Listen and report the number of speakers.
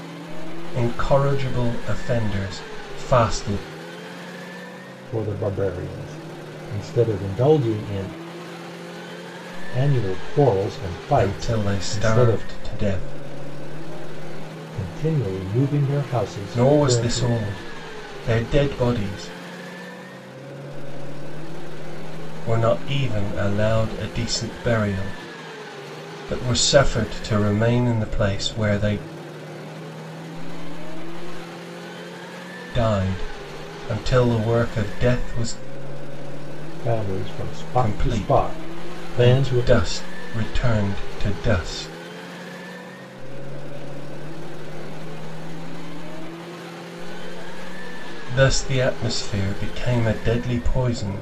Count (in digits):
3